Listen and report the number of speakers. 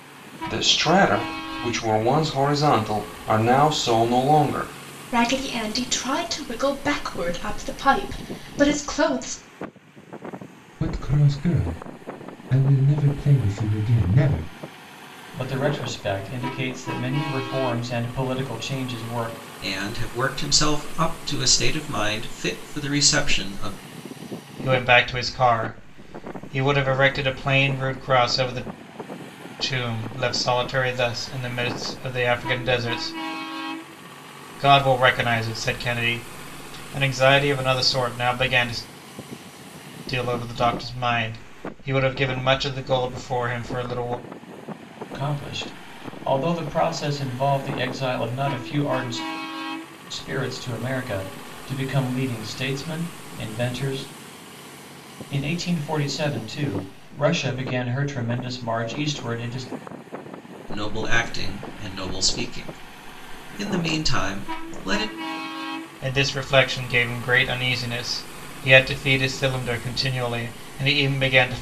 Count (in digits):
6